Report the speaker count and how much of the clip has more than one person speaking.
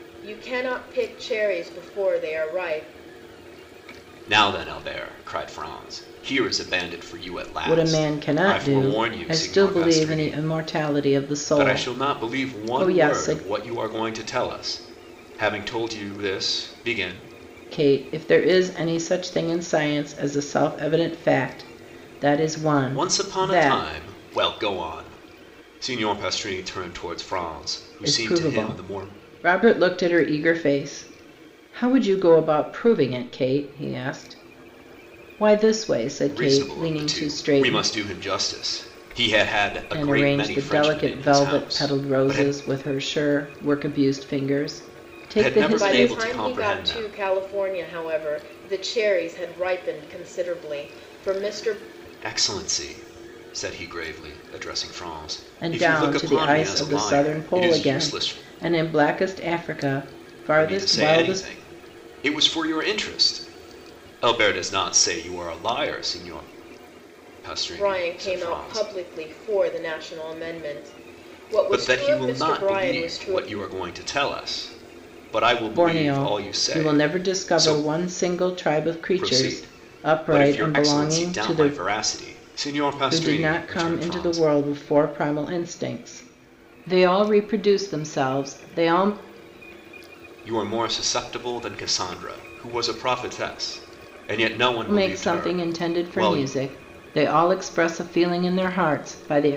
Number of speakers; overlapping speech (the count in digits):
3, about 28%